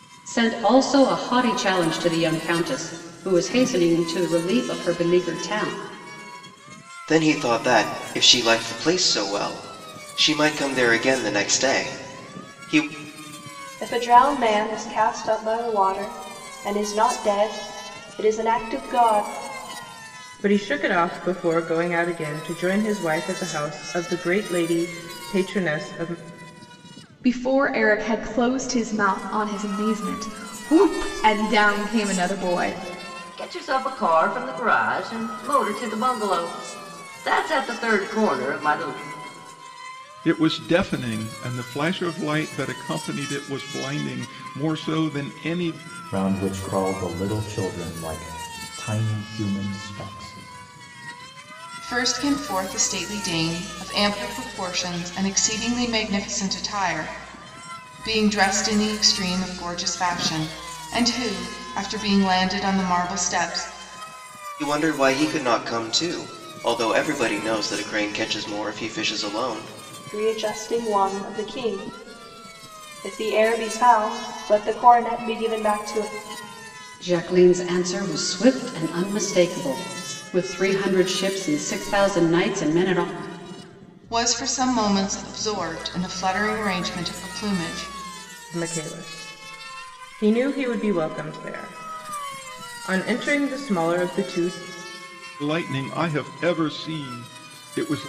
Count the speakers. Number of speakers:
nine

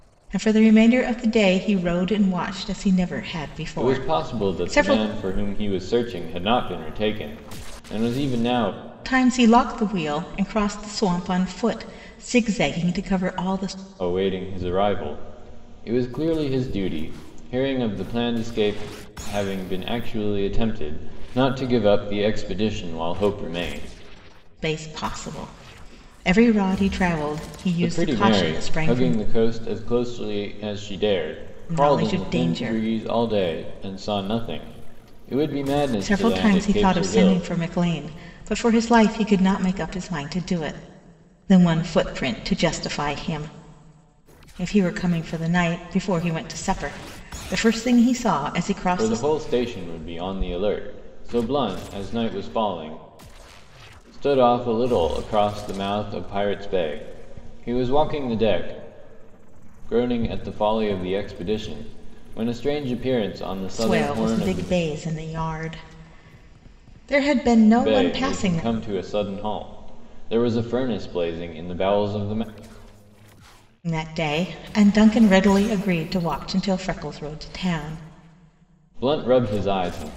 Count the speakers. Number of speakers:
two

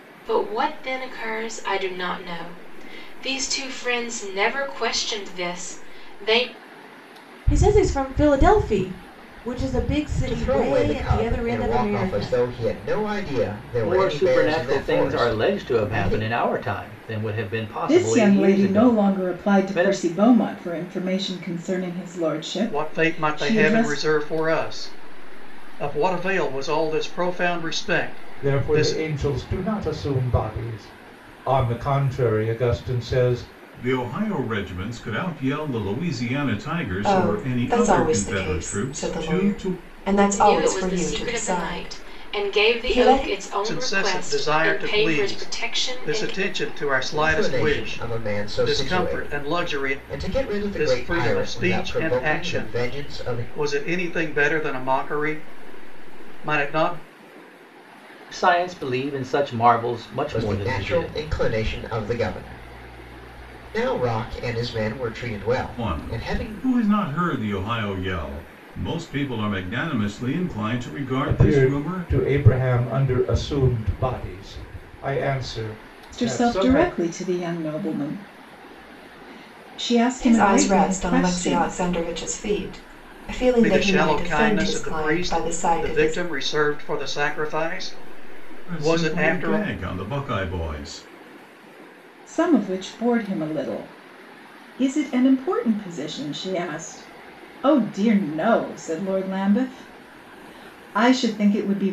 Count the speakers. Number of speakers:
nine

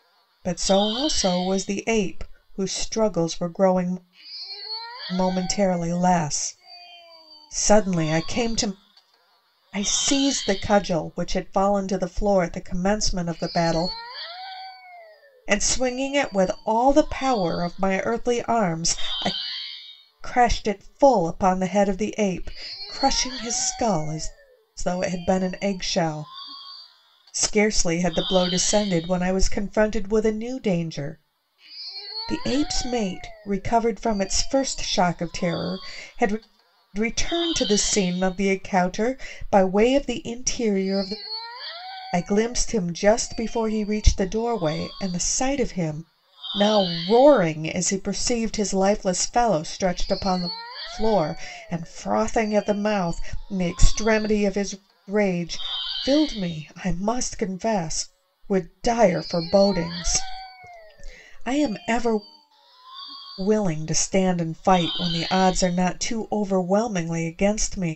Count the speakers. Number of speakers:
one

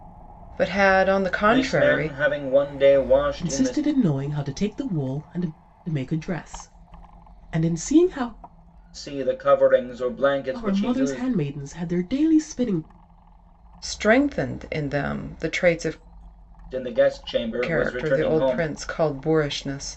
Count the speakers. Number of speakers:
three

